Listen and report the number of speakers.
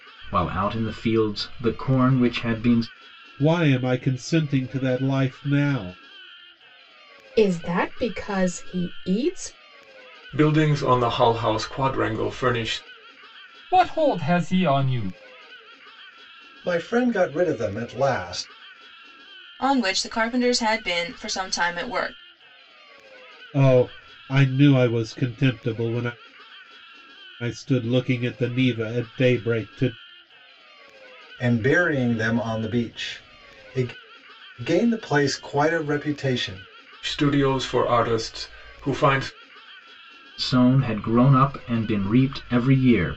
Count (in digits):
7